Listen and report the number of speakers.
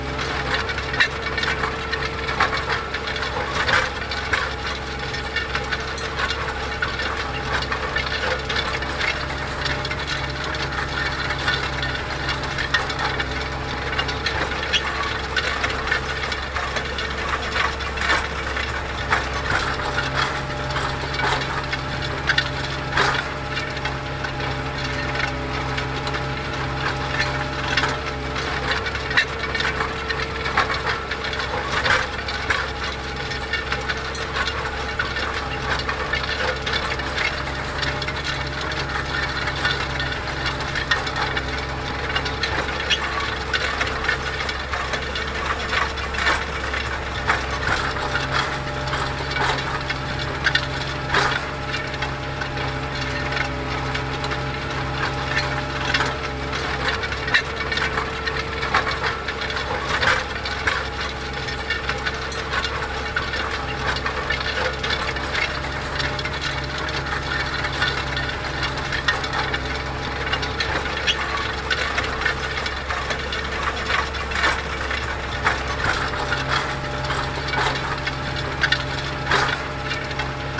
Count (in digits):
0